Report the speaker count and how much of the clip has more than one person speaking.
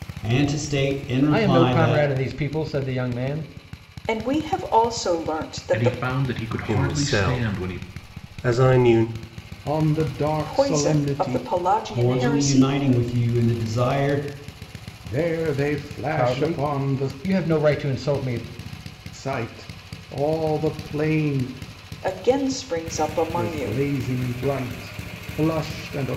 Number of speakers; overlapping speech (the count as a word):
six, about 22%